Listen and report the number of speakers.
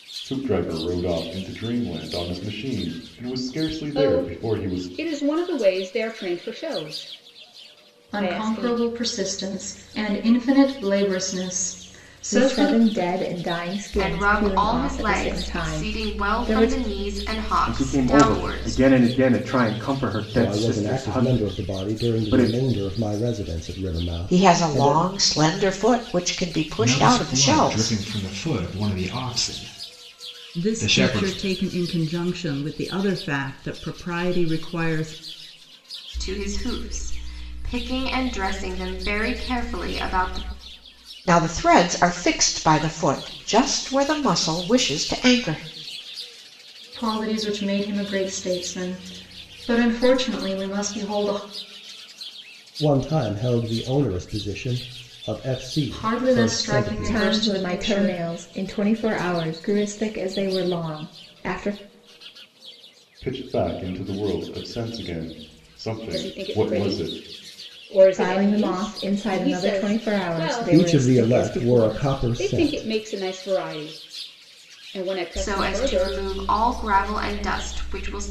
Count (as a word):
ten